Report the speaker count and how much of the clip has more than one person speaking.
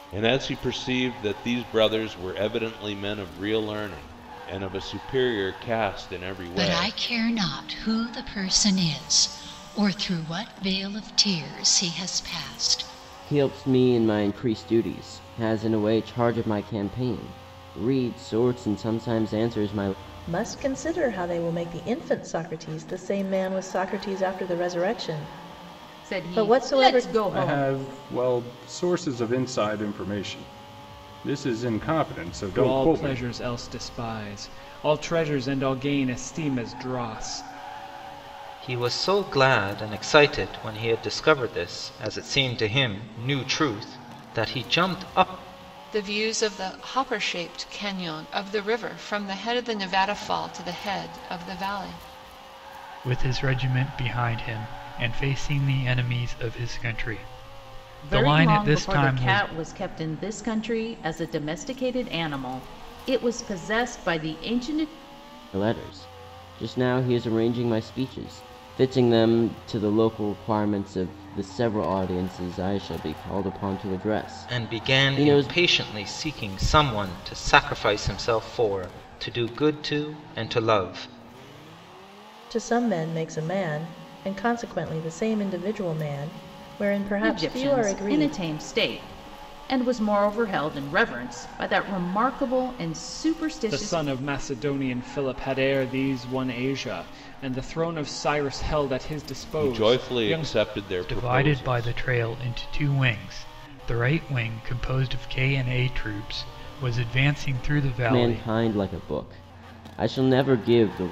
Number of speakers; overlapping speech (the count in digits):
10, about 8%